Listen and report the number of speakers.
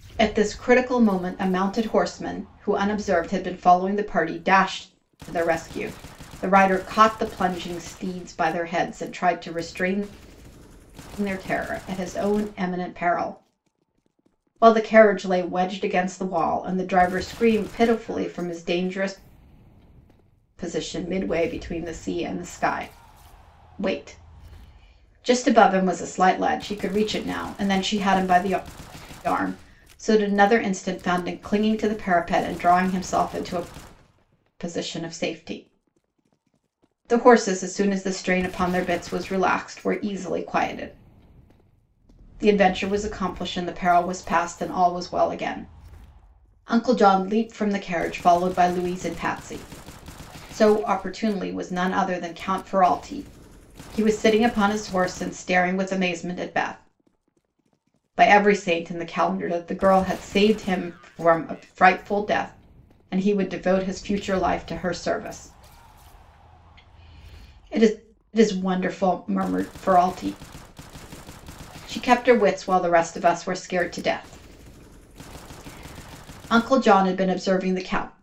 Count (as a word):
one